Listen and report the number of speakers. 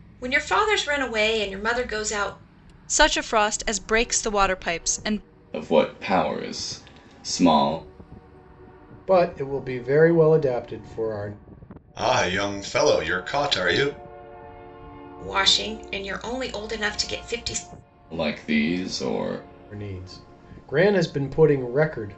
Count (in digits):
5